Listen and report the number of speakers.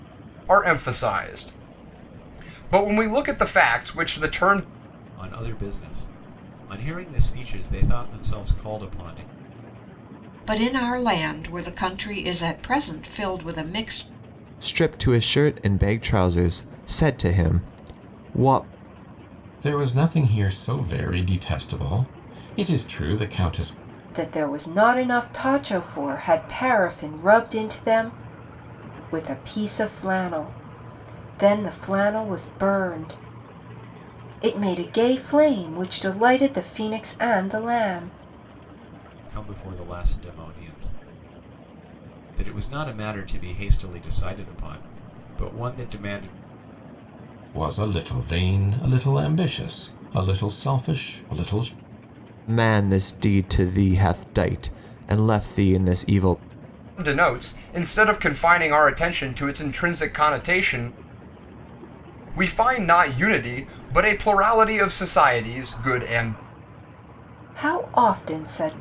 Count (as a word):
six